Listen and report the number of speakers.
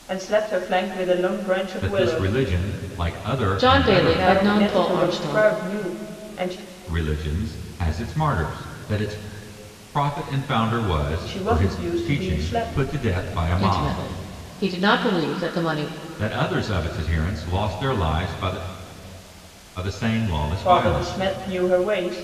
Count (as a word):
three